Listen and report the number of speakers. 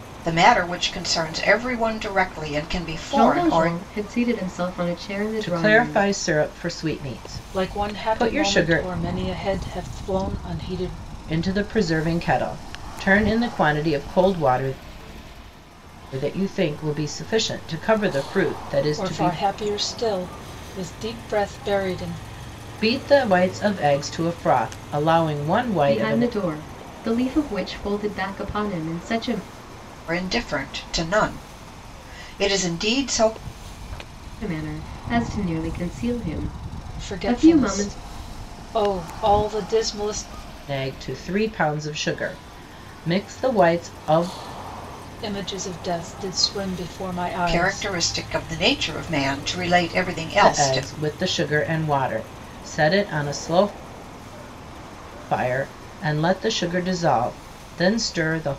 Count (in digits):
4